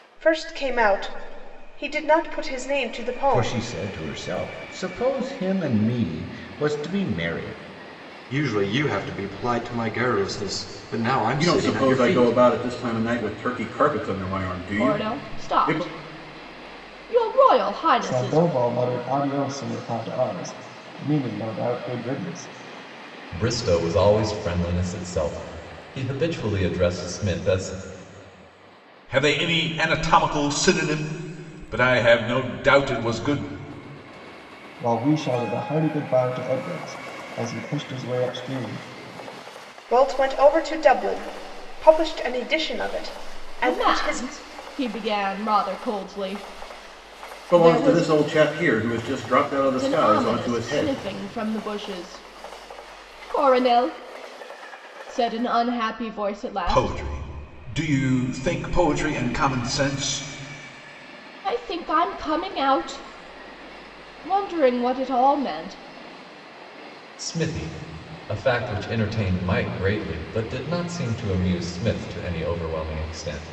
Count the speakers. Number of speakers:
8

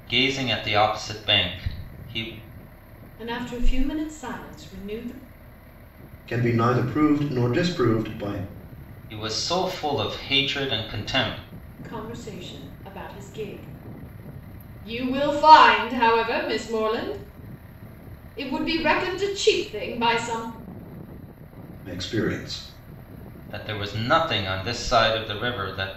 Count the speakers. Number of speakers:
3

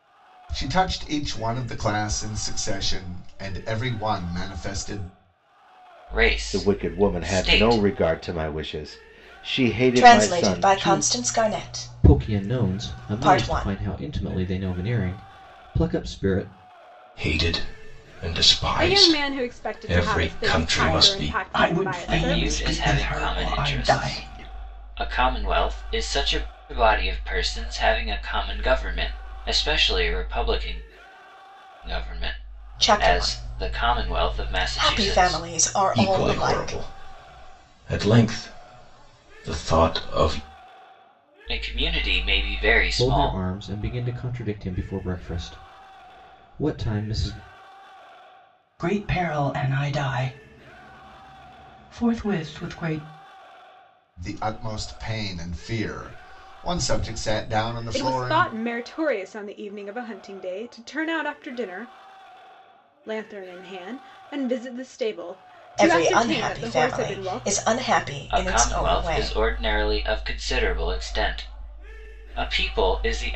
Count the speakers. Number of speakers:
8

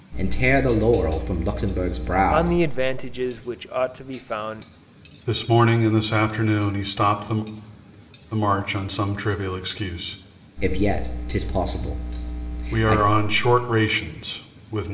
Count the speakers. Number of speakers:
3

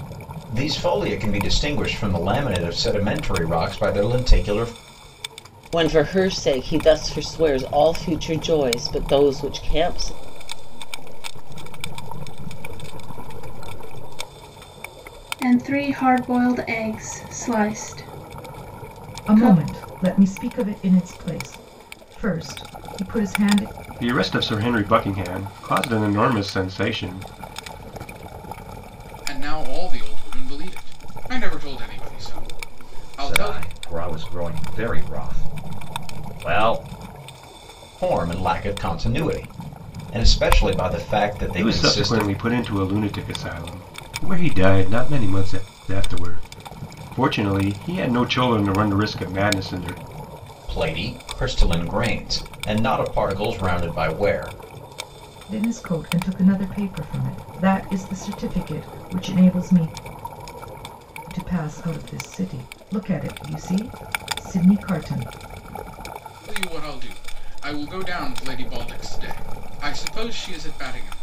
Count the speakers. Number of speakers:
8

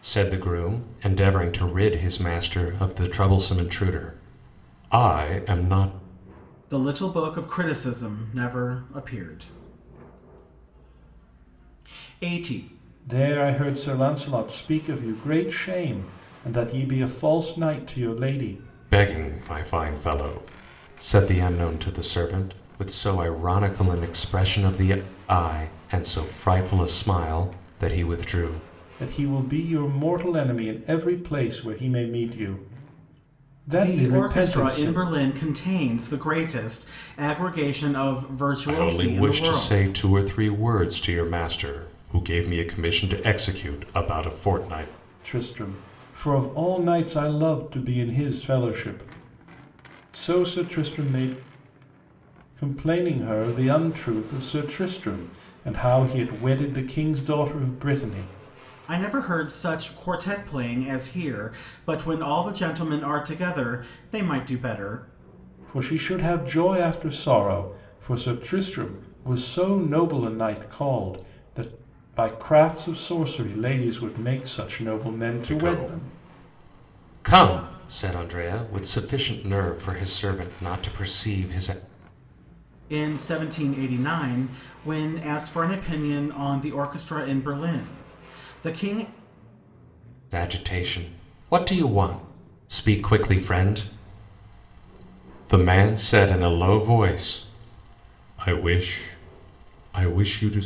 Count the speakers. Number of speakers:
3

